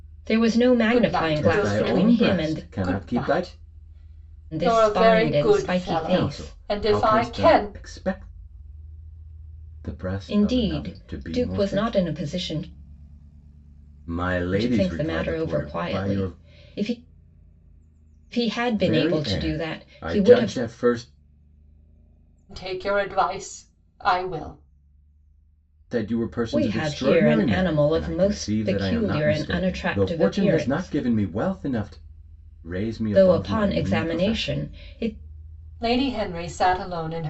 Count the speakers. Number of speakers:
3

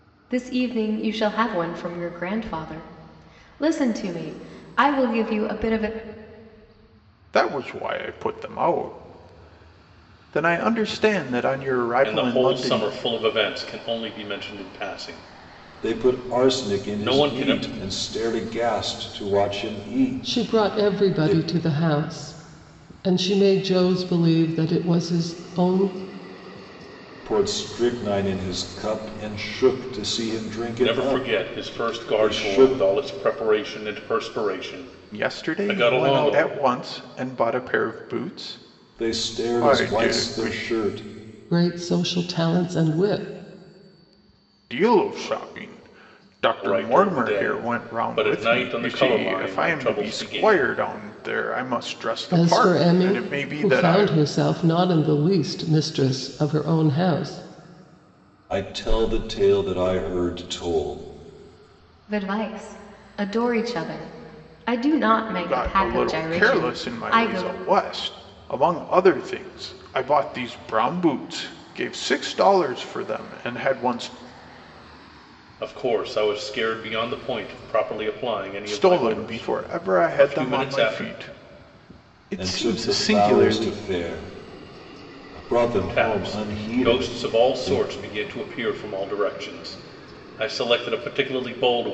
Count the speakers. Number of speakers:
5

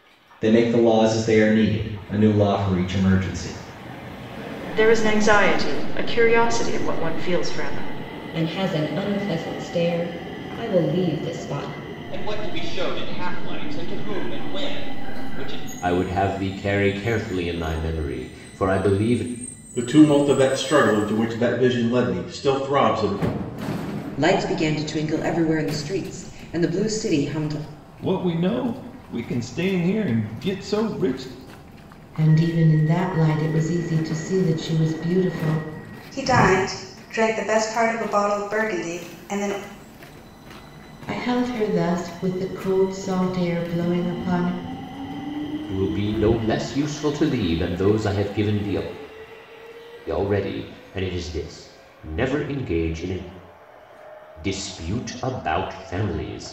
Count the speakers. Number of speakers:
10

